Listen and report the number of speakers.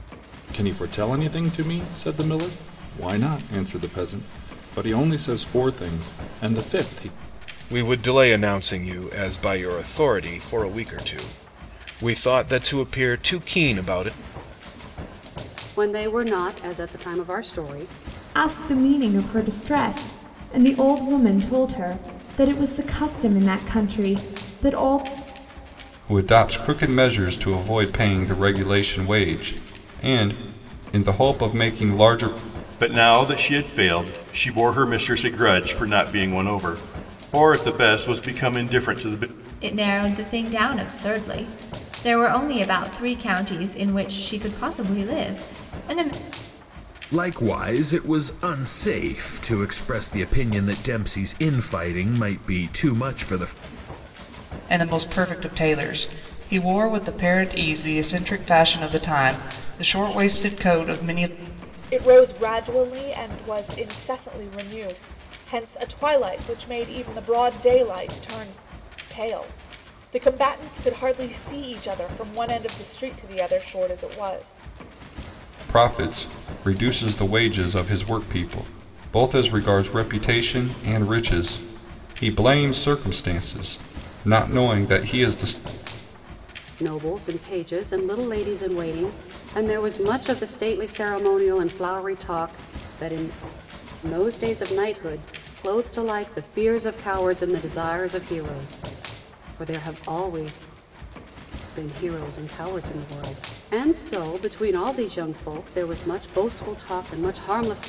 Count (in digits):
10